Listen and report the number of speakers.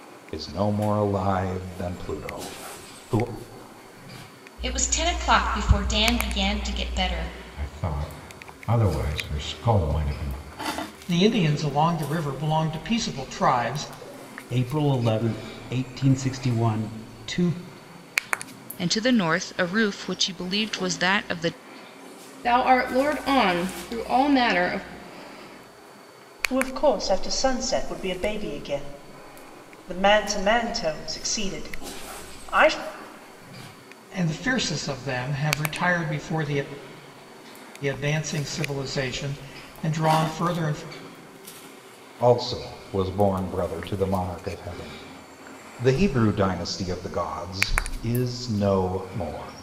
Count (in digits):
8